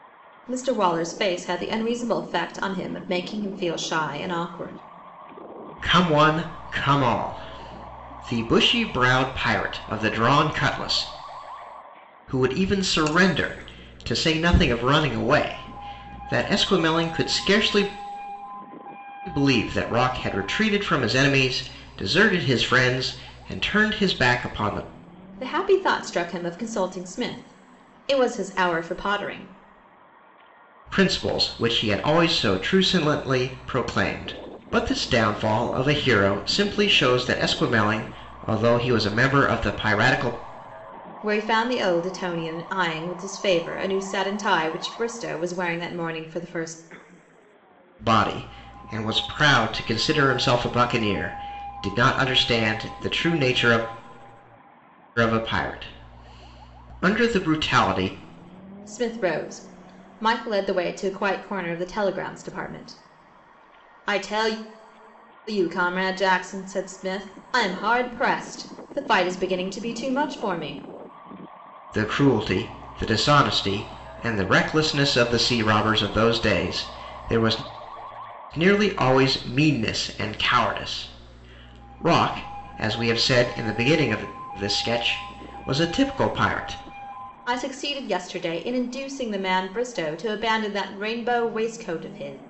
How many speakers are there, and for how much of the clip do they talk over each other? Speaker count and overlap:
2, no overlap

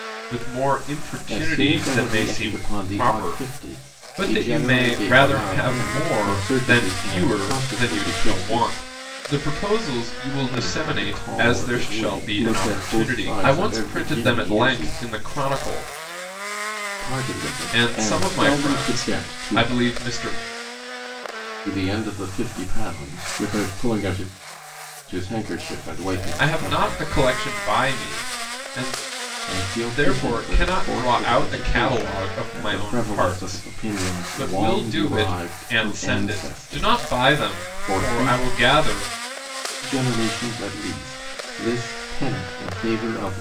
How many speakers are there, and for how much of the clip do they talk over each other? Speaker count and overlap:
2, about 51%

